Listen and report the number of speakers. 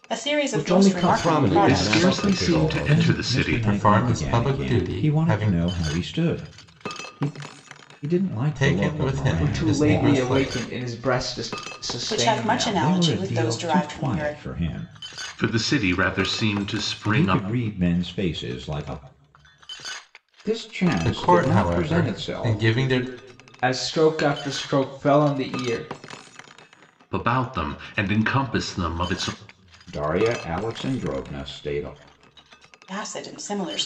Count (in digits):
6